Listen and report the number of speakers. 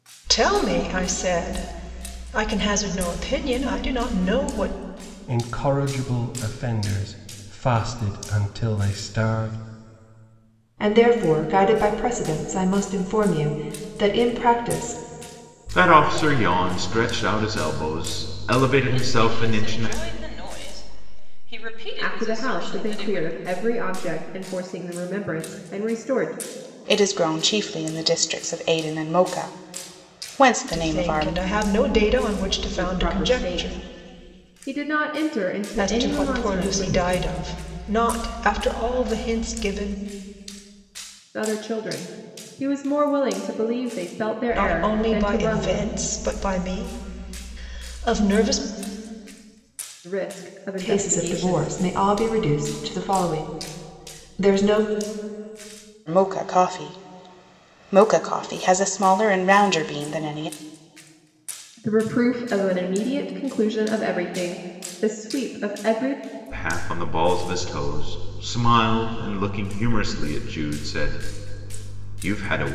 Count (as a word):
seven